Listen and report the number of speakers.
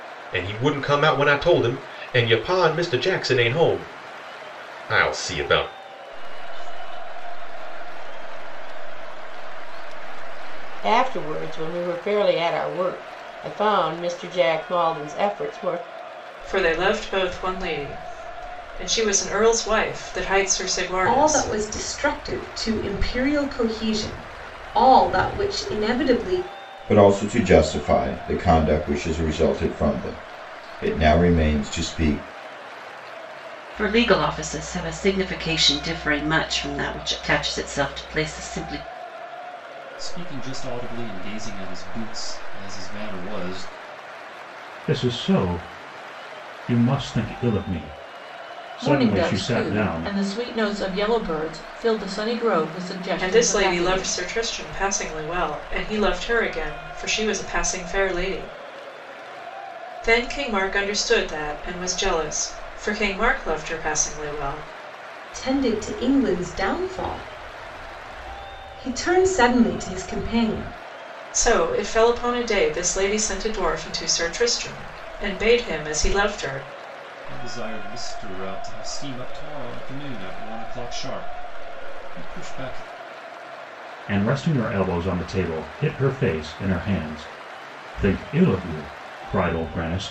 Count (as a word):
ten